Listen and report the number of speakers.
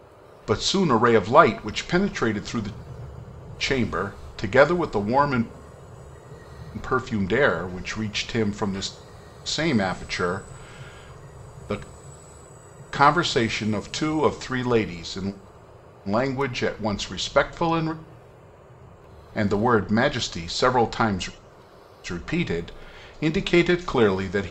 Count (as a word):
one